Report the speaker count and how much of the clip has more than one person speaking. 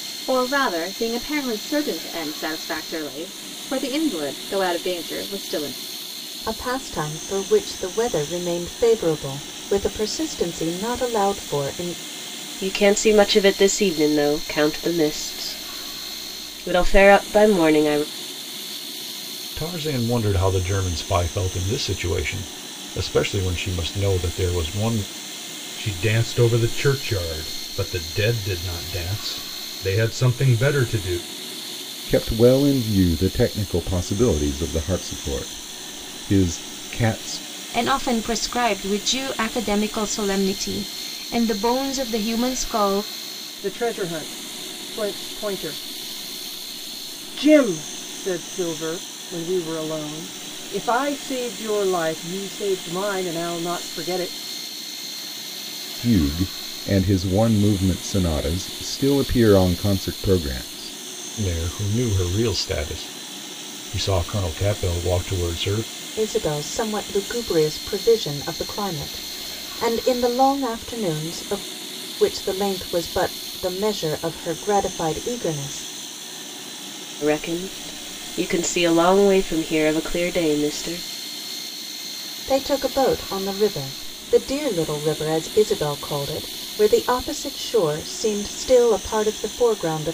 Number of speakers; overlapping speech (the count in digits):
8, no overlap